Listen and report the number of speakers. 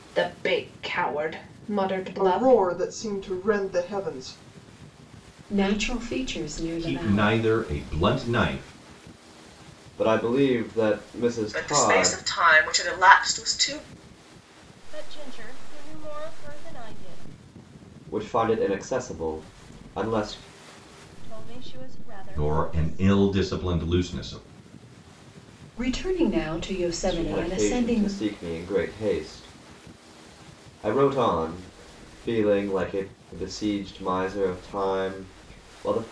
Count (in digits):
7